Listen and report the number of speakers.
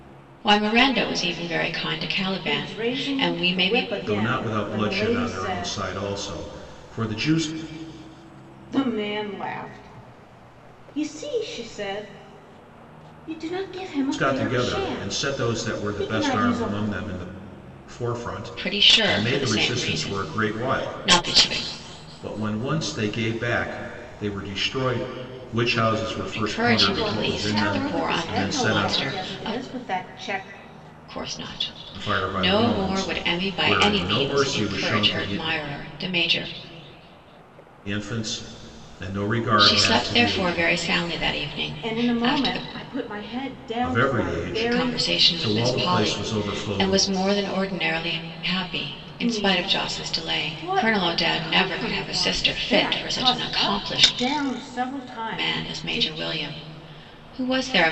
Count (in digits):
3